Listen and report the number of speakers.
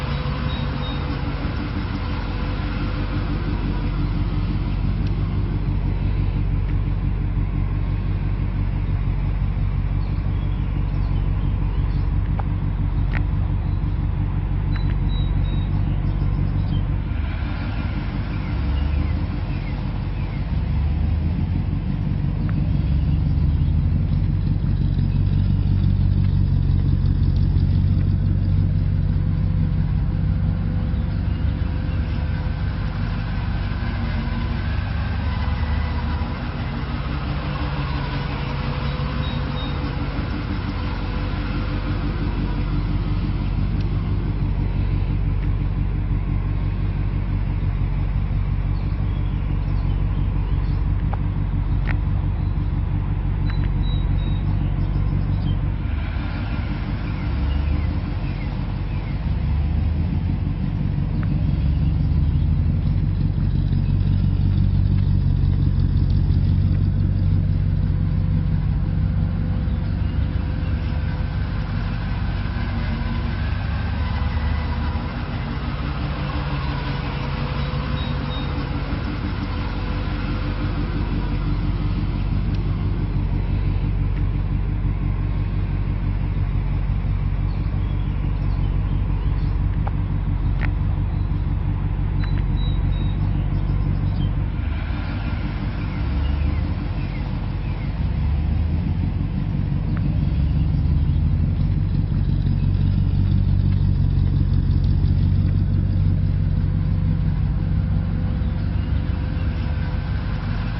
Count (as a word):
zero